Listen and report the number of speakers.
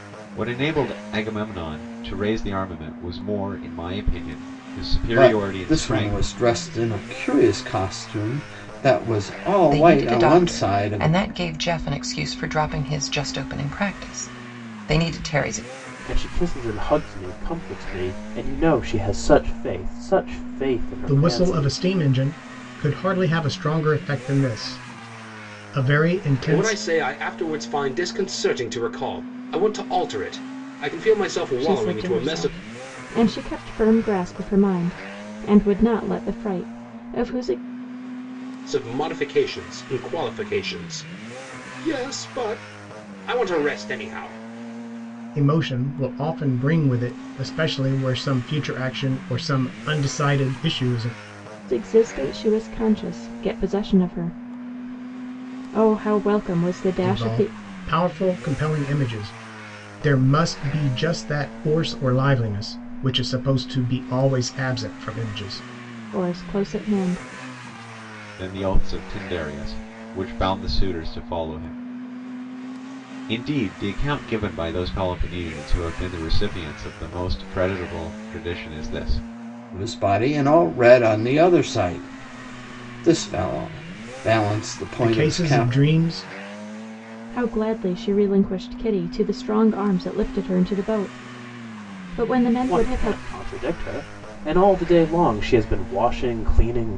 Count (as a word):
seven